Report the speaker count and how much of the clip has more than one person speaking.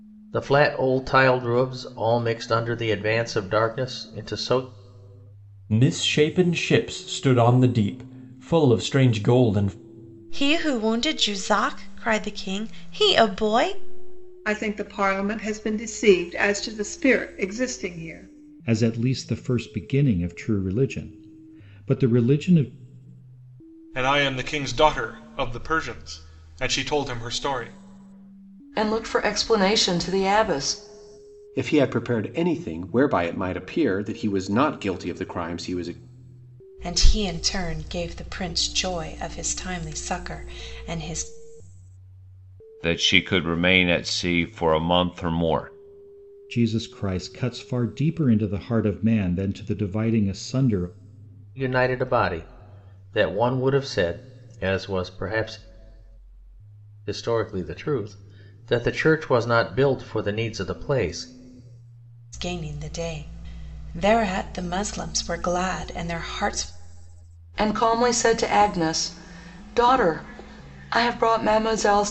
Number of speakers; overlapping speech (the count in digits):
10, no overlap